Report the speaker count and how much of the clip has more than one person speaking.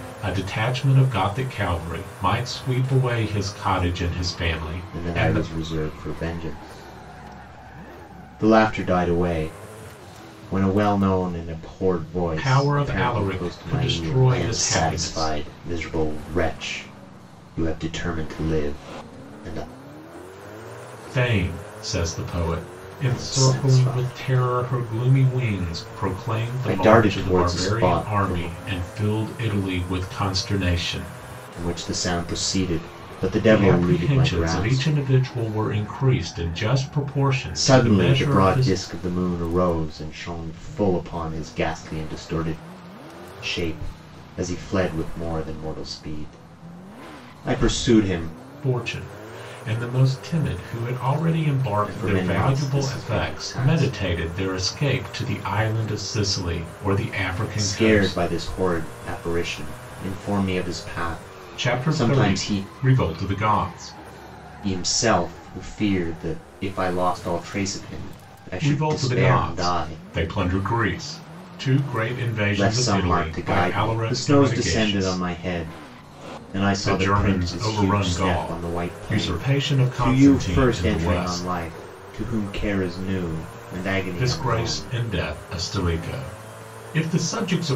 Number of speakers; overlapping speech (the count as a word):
two, about 29%